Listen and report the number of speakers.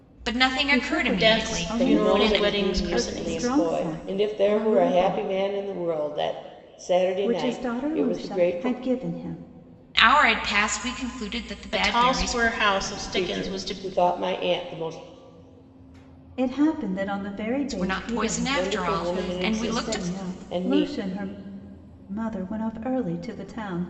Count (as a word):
four